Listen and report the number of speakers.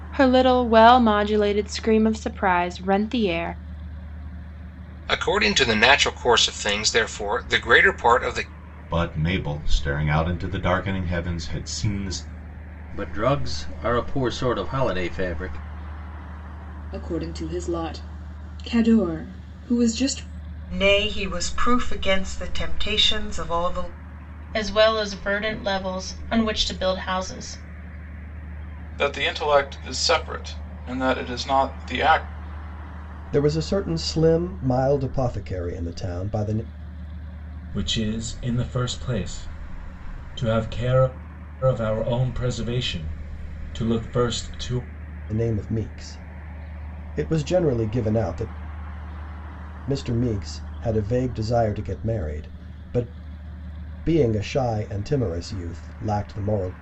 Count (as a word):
ten